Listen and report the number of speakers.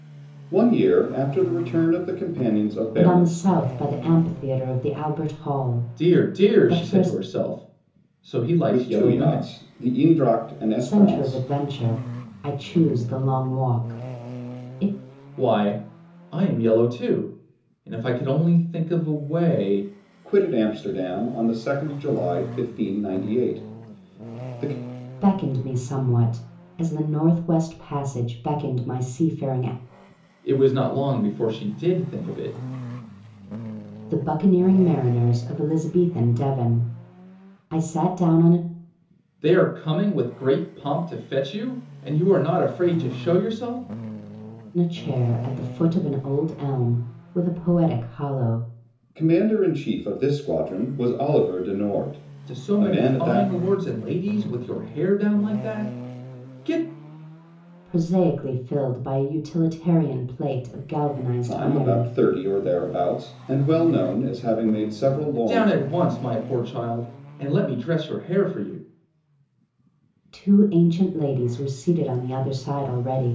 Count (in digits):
3